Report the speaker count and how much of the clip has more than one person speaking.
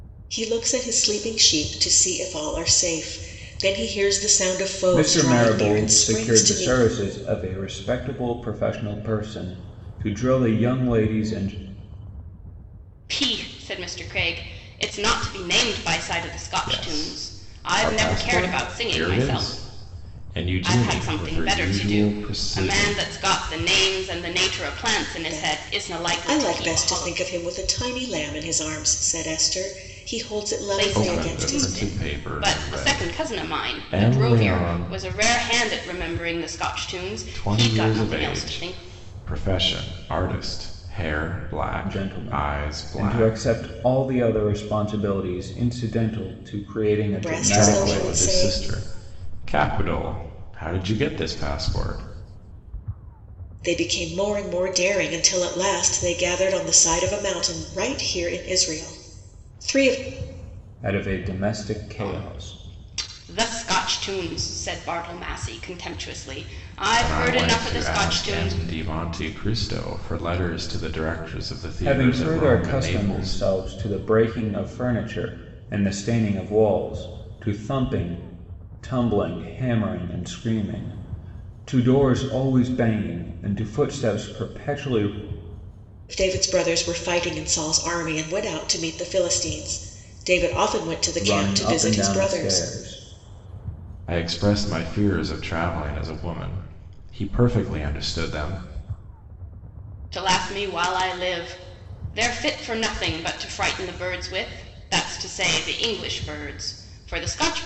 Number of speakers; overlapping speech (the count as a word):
four, about 22%